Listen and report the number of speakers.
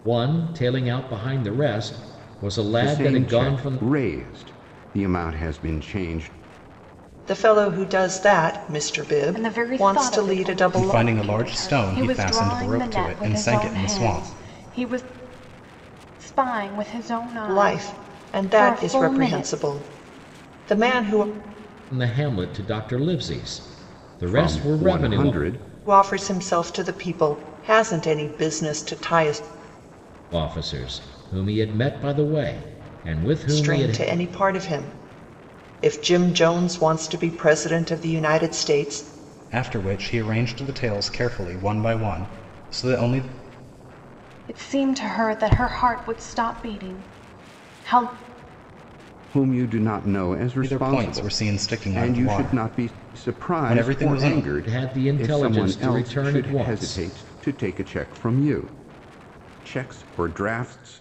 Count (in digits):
5